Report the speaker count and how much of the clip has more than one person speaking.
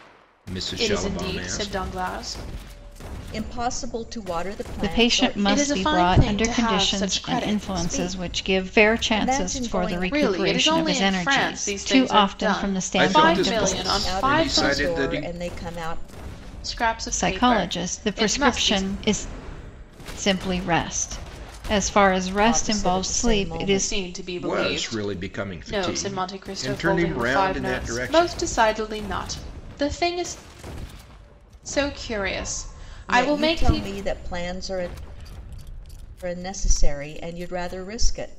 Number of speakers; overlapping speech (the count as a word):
four, about 50%